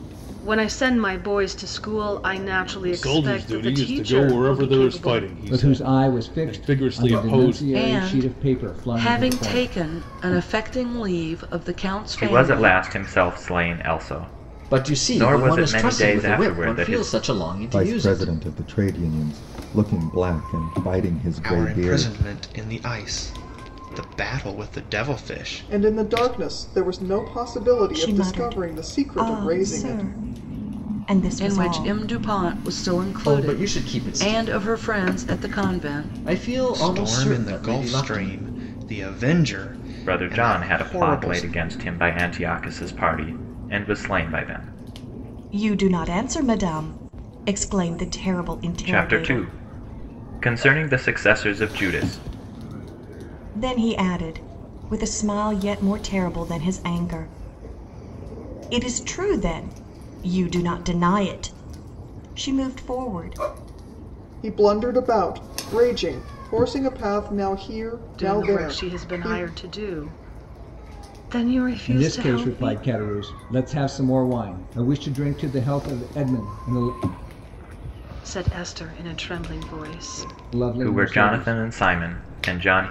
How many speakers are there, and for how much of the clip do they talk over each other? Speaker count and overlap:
10, about 30%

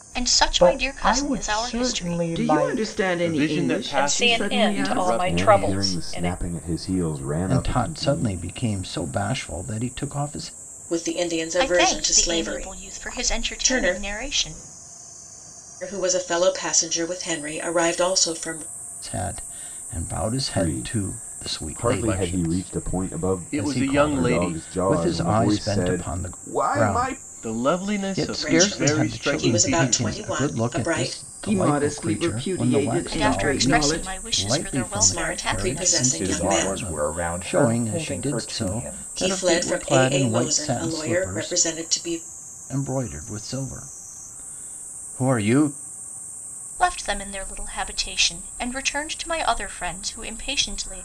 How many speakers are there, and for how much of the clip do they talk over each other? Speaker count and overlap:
8, about 58%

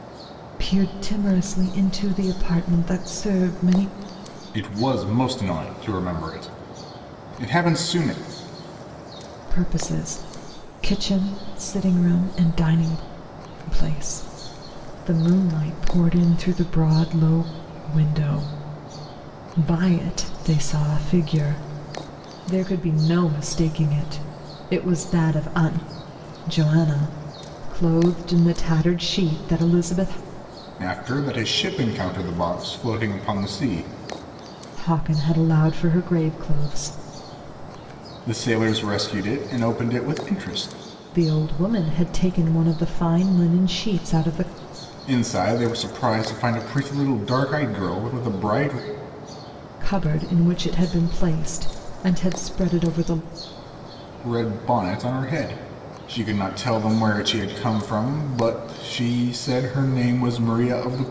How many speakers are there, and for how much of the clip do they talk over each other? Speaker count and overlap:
2, no overlap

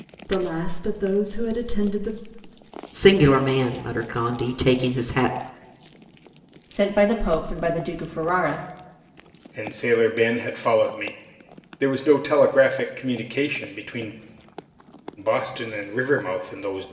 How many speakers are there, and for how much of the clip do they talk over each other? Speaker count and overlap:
4, no overlap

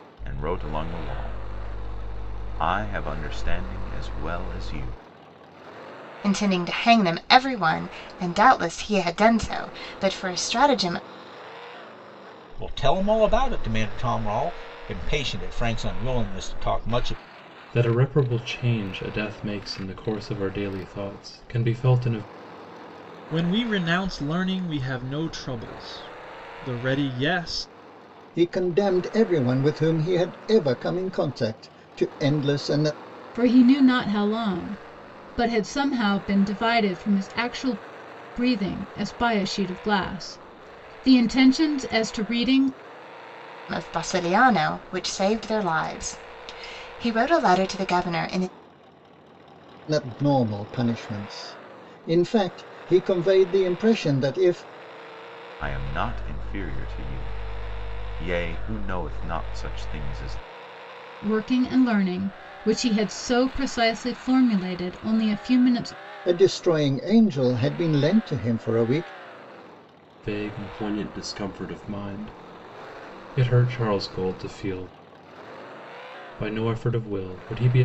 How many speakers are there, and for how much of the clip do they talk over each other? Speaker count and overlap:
7, no overlap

